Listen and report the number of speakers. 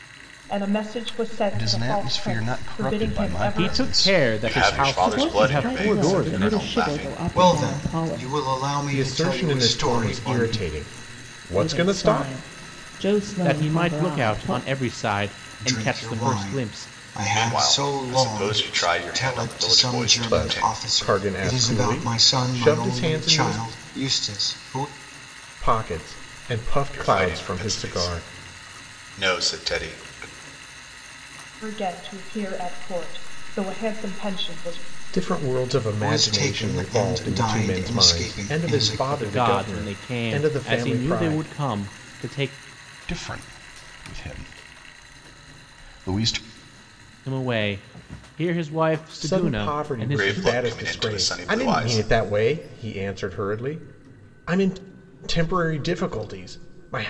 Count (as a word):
seven